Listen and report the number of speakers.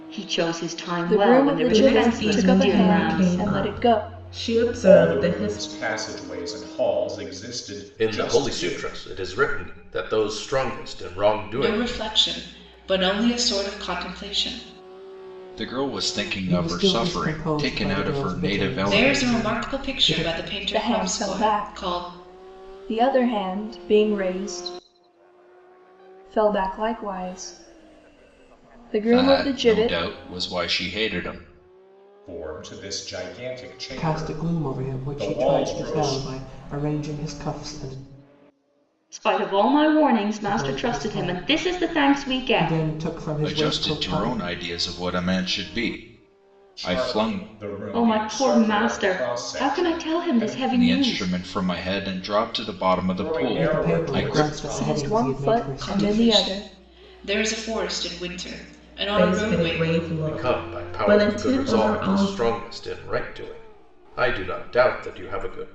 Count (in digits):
8